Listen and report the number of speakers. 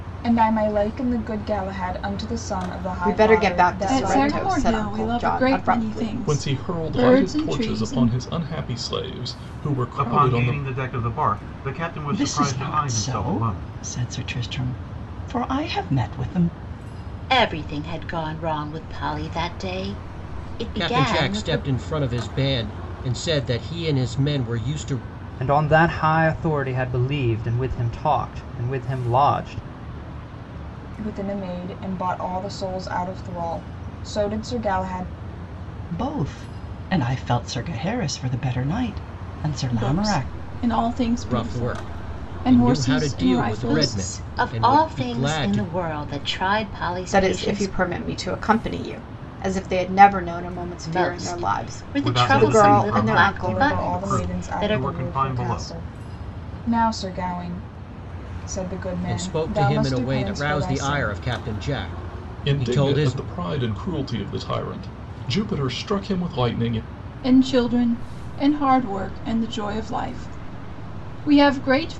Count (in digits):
9